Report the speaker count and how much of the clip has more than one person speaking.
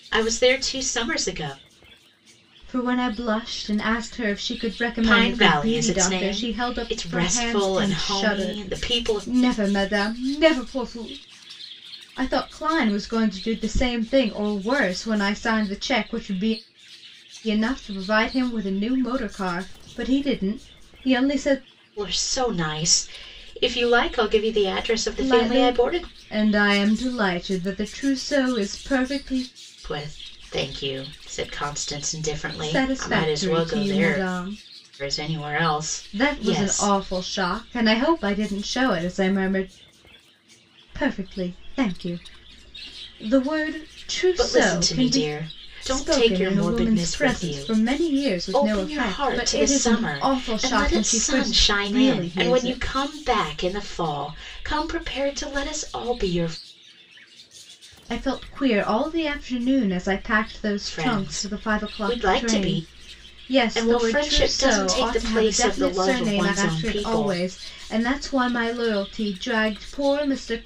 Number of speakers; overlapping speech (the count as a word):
two, about 29%